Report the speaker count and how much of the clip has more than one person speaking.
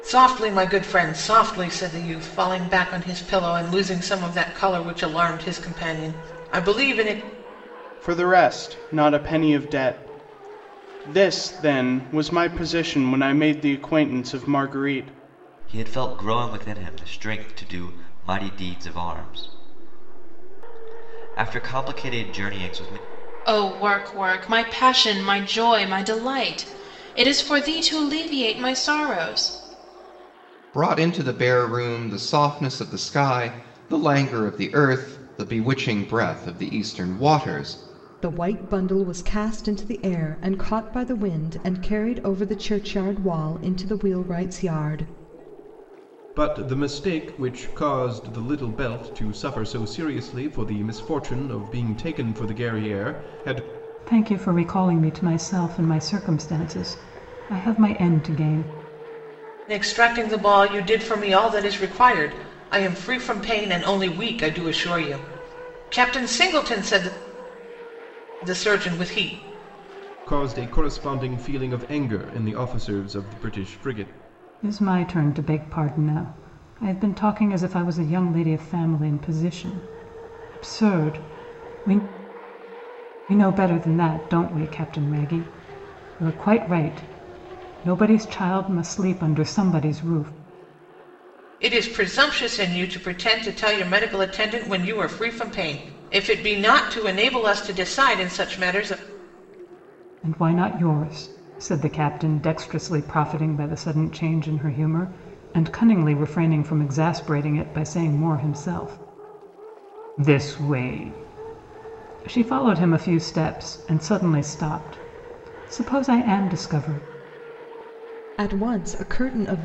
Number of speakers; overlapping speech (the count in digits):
8, no overlap